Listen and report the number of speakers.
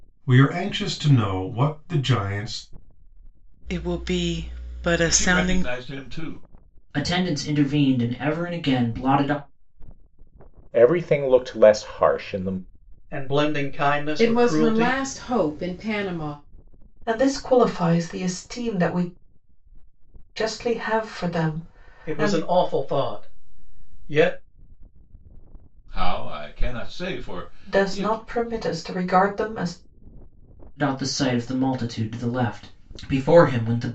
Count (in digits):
8